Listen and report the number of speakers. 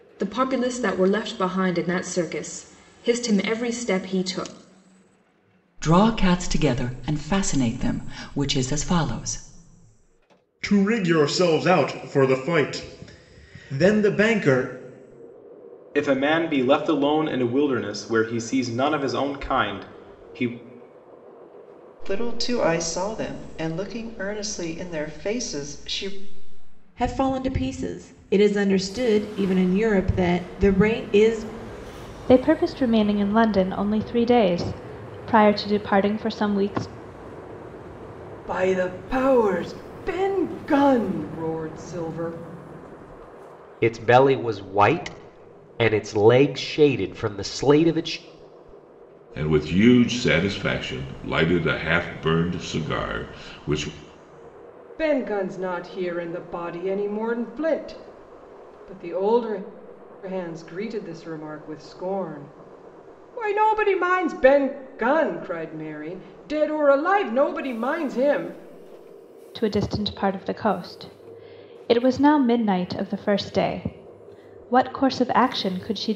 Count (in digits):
10